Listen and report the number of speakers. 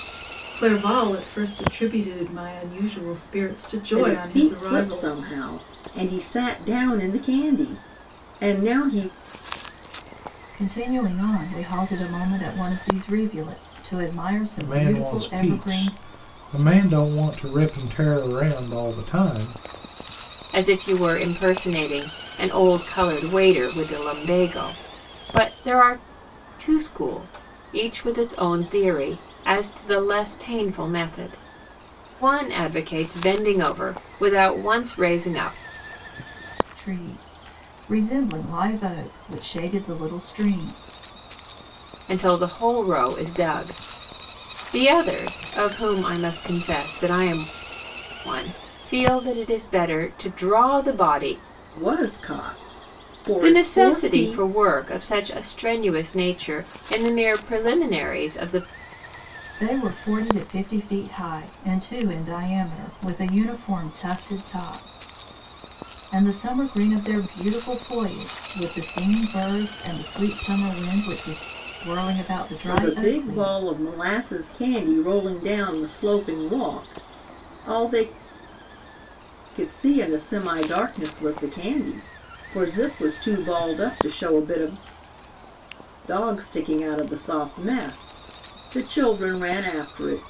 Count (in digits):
5